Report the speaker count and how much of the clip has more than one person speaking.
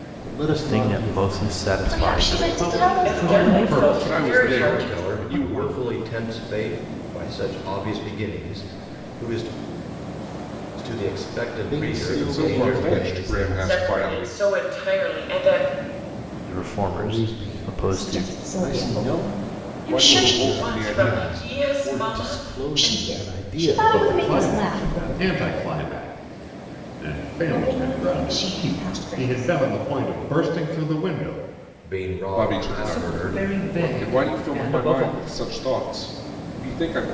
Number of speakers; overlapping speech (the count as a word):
eight, about 56%